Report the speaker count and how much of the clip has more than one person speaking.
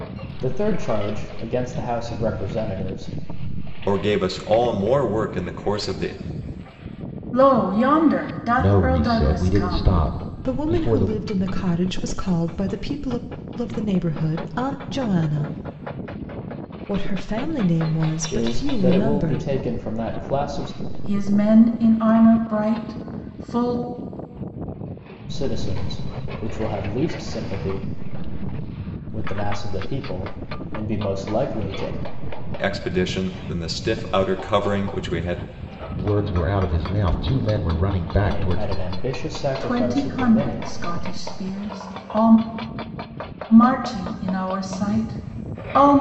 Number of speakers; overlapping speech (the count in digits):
5, about 11%